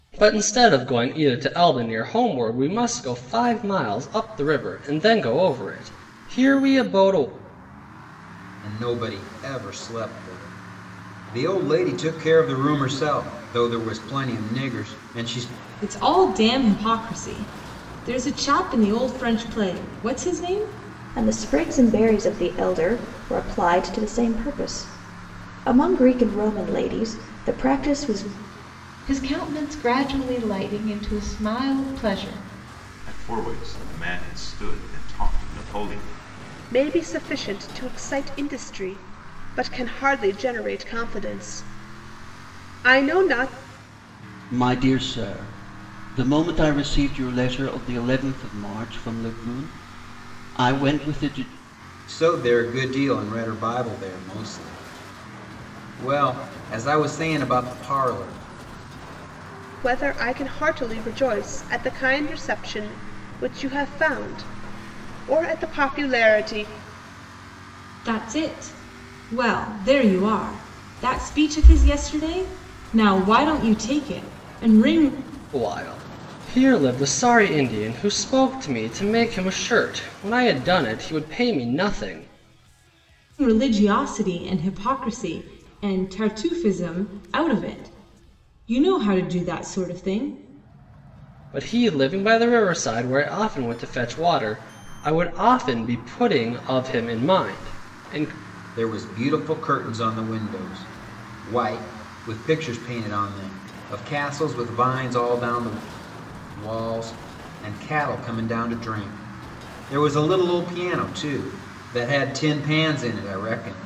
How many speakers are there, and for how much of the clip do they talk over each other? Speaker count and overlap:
8, no overlap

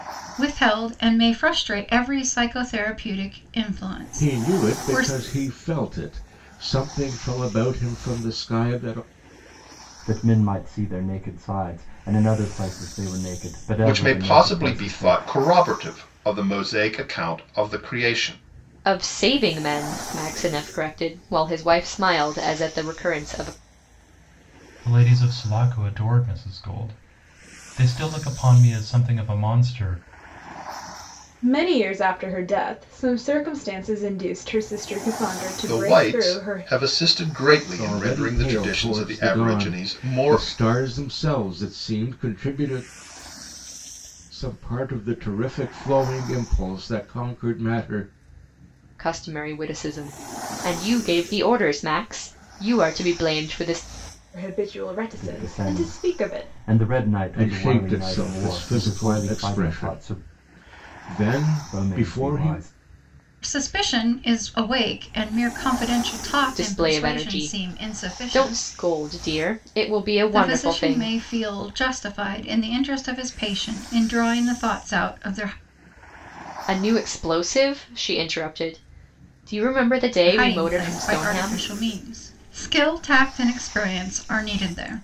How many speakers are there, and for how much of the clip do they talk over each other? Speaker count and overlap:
7, about 19%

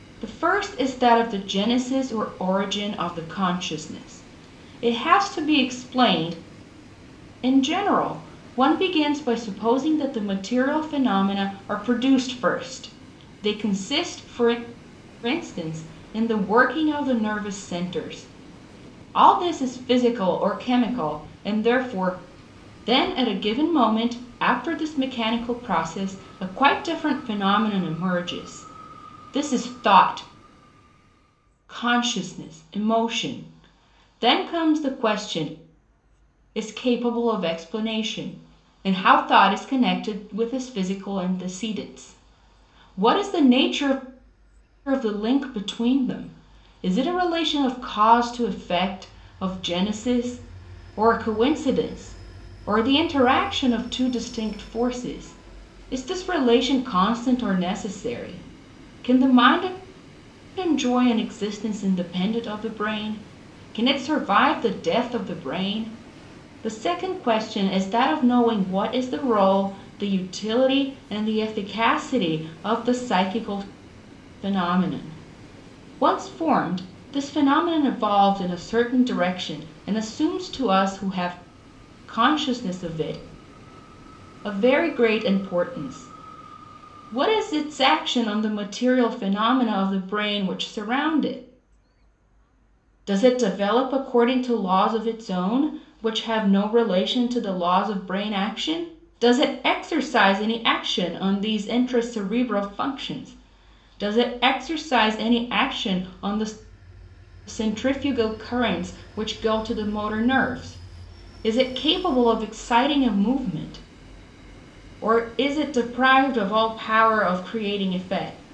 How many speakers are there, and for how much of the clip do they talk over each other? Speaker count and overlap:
1, no overlap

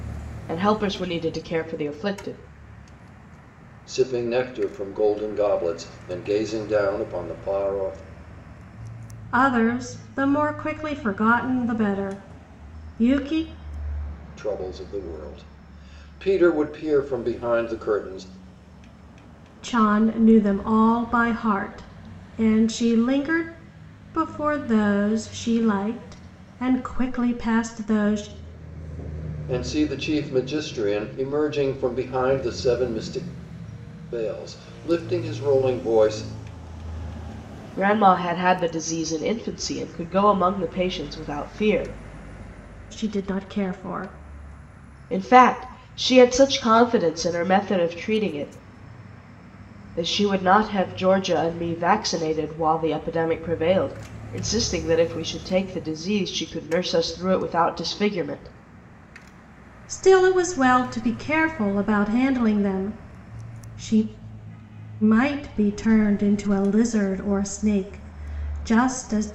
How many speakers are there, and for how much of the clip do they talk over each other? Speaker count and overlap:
3, no overlap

